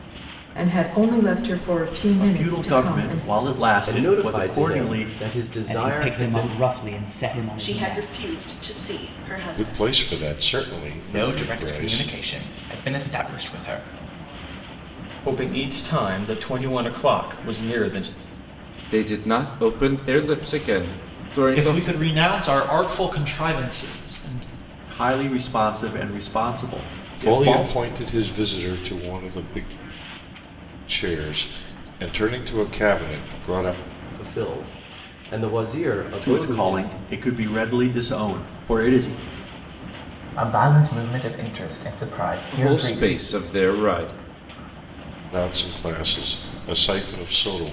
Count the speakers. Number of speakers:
10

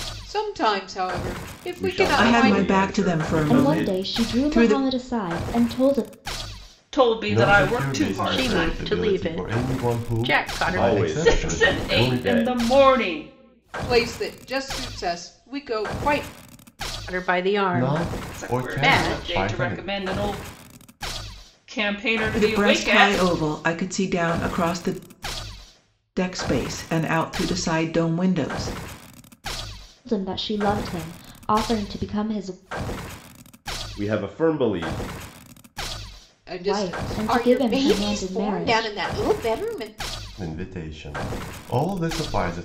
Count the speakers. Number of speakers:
7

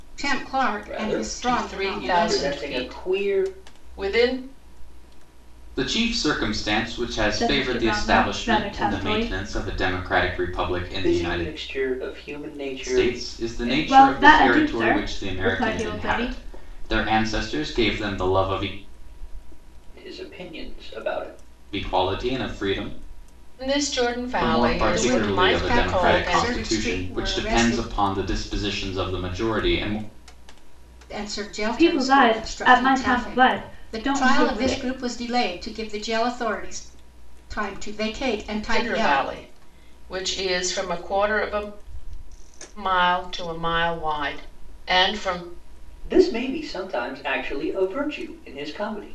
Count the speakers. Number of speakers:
5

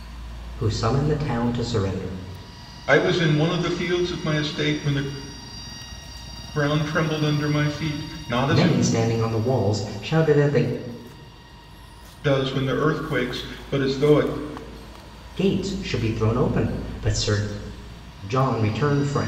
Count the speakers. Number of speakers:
2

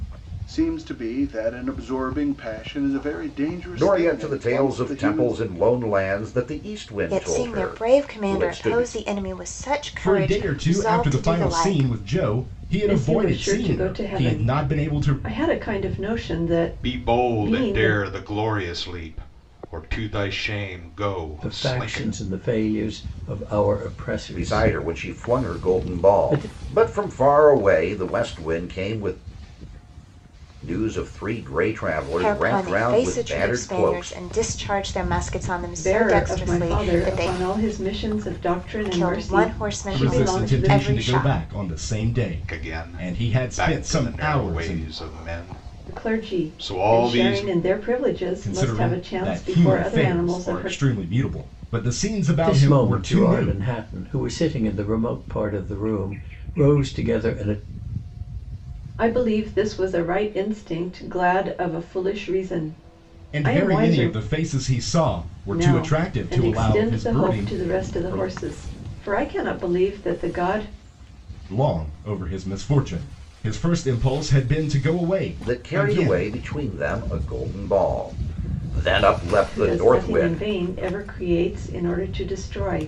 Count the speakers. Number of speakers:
7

